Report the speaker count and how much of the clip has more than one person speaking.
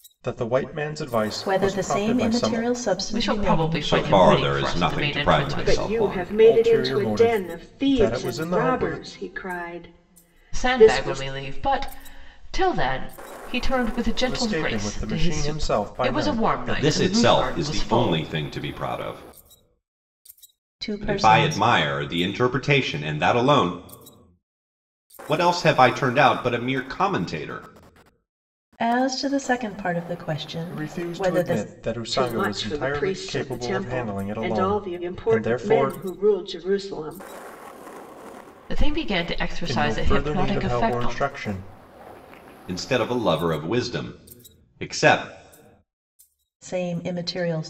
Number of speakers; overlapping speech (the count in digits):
5, about 39%